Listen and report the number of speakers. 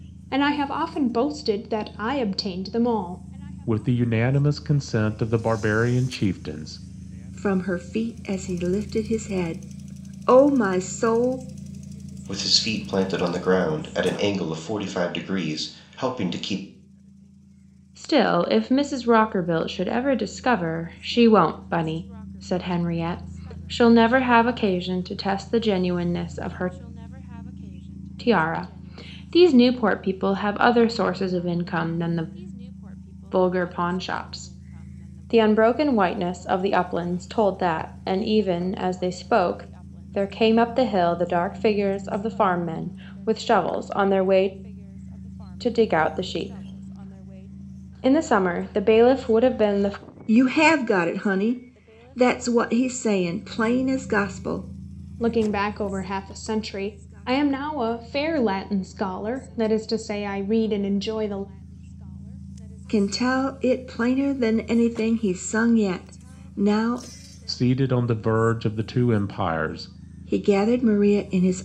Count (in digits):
5